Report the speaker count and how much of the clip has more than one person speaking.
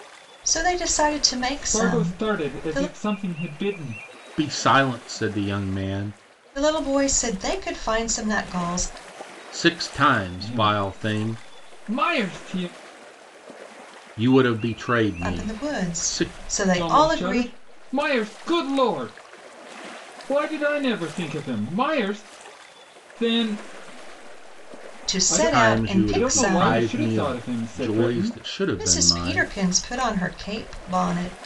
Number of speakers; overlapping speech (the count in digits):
3, about 26%